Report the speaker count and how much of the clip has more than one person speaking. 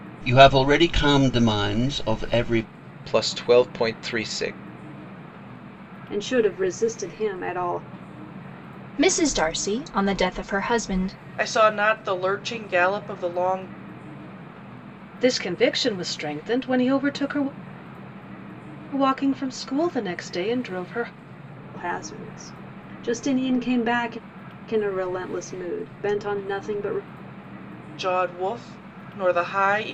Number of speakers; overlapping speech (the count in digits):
6, no overlap